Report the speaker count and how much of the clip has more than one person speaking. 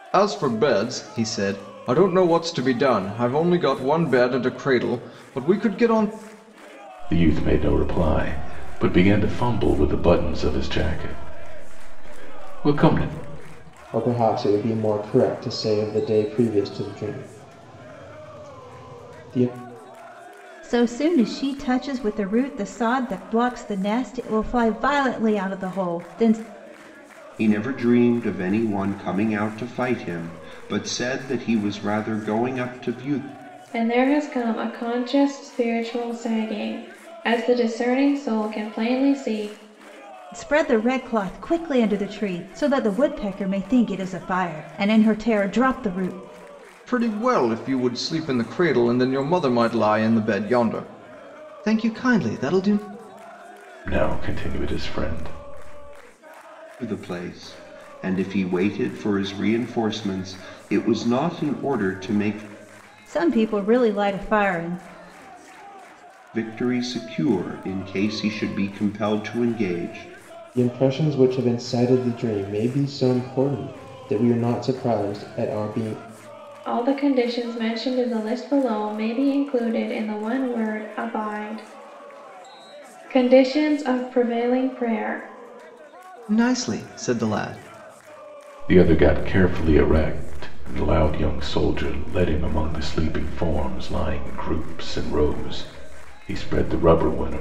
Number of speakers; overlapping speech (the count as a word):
six, no overlap